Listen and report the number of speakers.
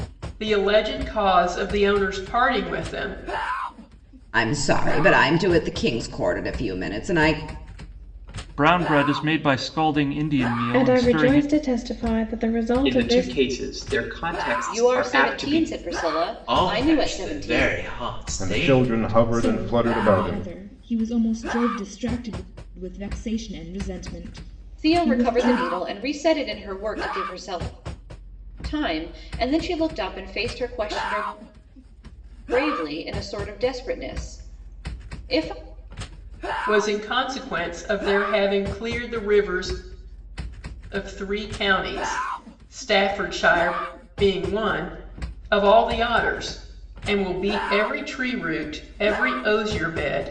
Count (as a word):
nine